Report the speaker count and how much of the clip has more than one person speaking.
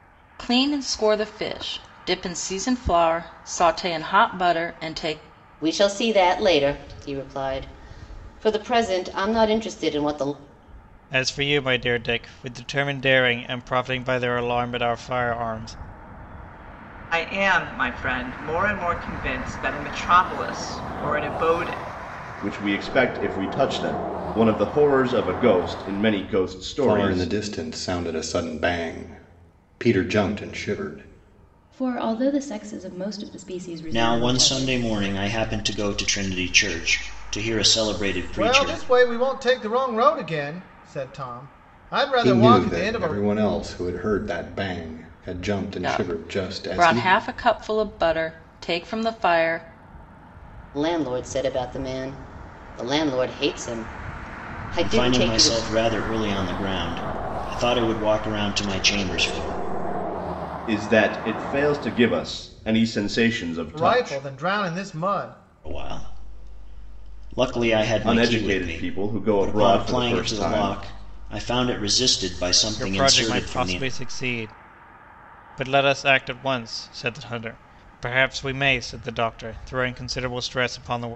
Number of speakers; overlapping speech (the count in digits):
9, about 11%